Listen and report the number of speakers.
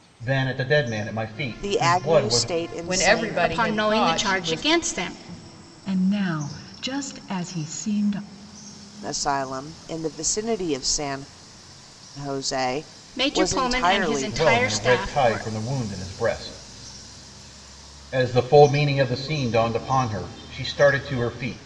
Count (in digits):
5